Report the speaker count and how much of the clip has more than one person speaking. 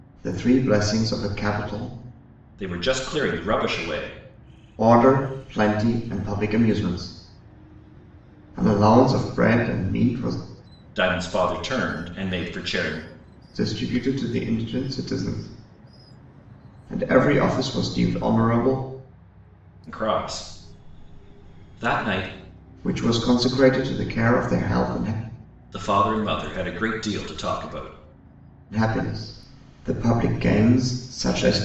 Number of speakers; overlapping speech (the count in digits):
2, no overlap